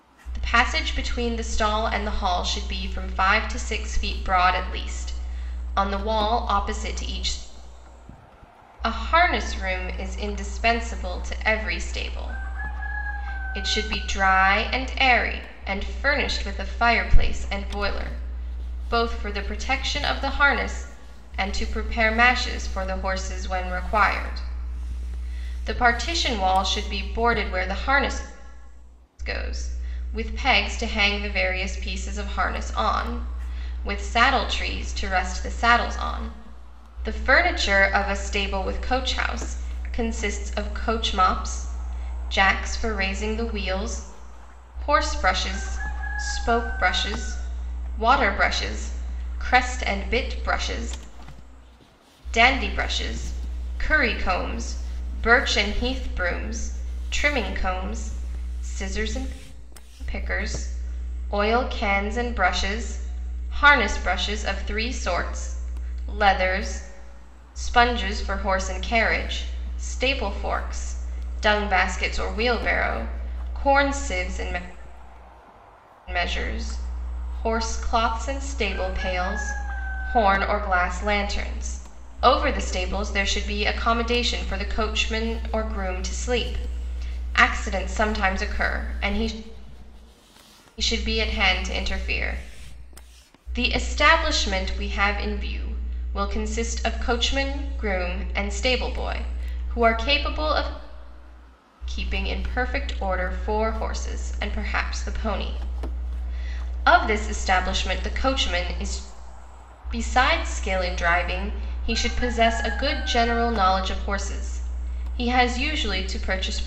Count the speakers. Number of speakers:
1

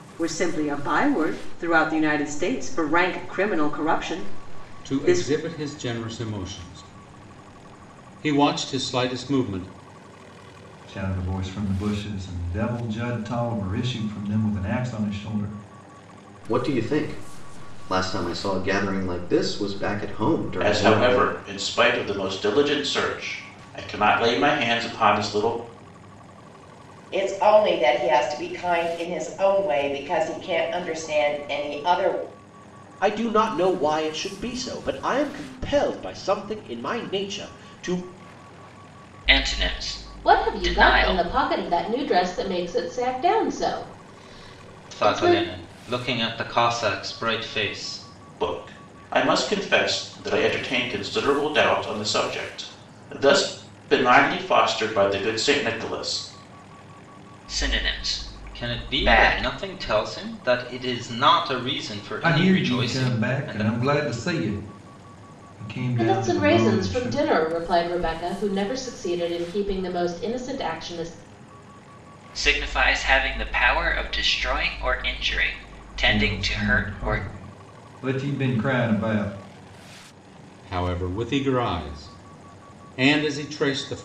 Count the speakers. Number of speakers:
10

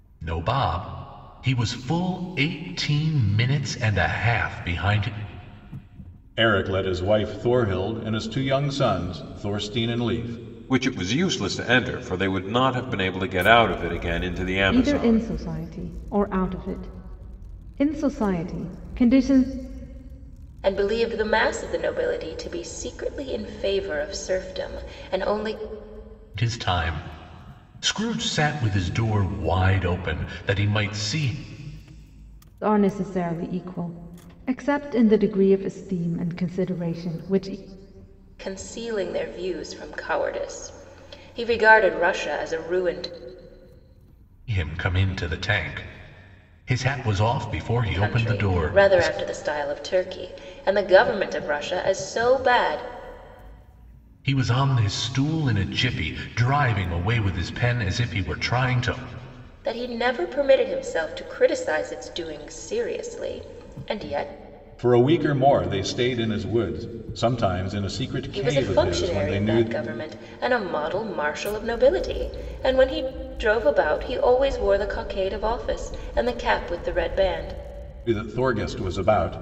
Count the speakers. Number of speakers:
5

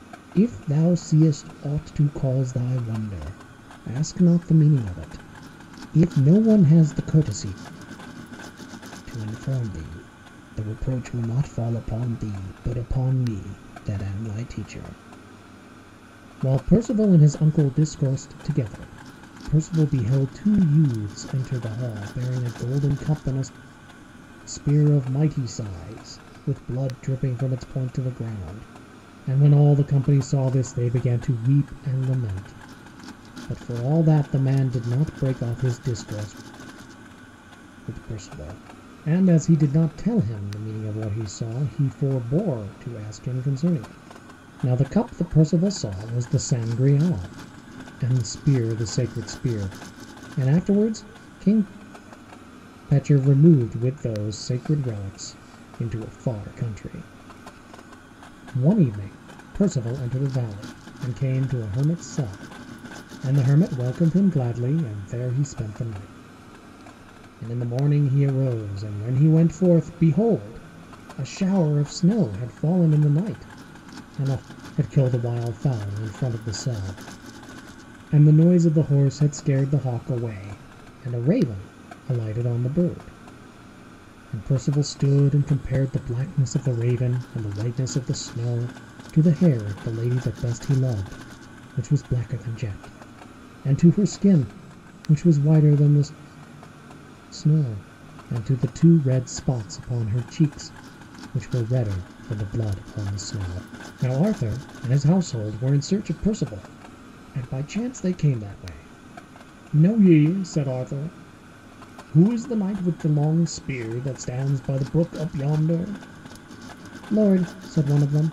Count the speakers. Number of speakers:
1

